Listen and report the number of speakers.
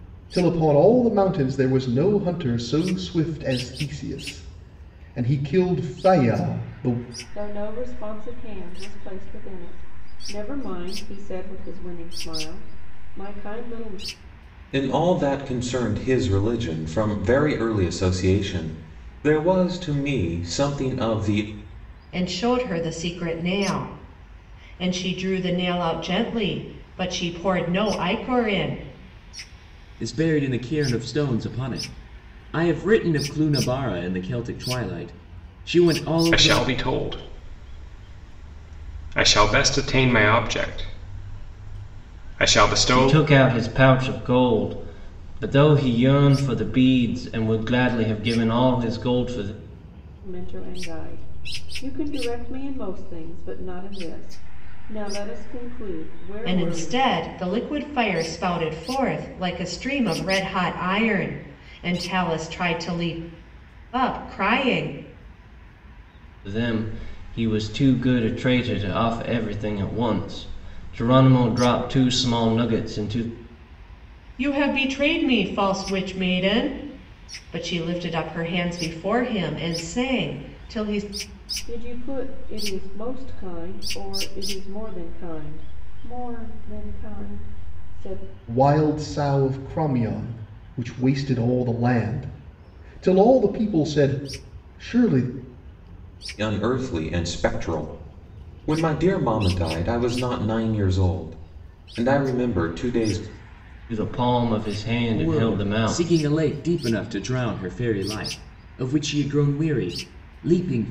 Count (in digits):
7